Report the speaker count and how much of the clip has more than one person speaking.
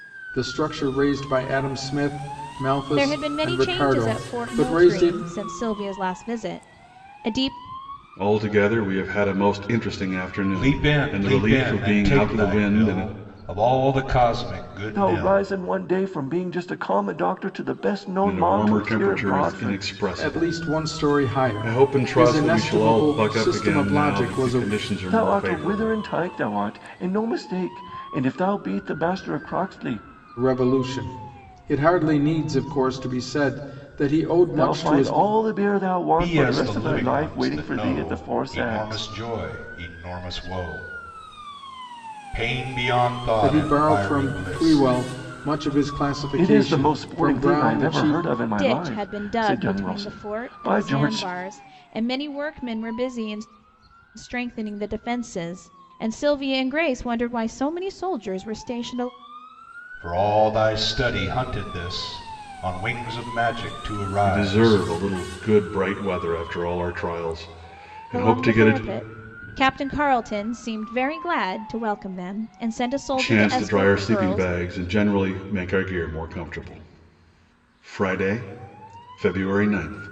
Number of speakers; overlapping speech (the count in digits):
5, about 31%